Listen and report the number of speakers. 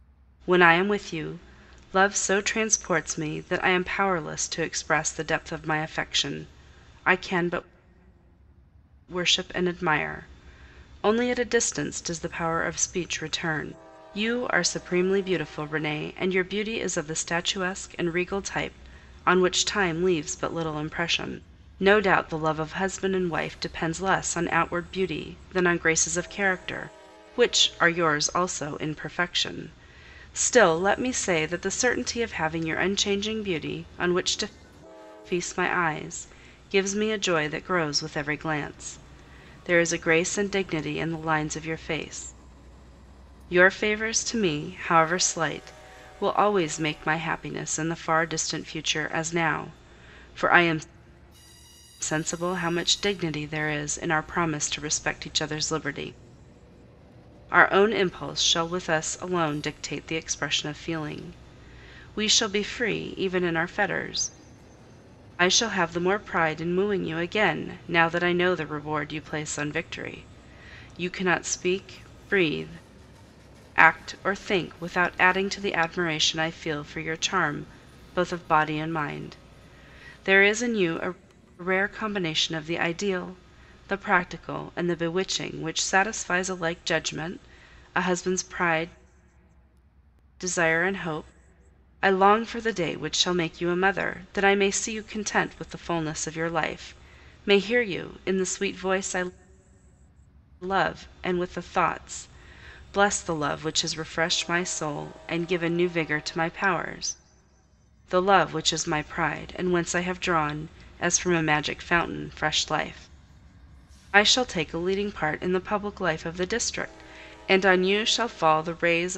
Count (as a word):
one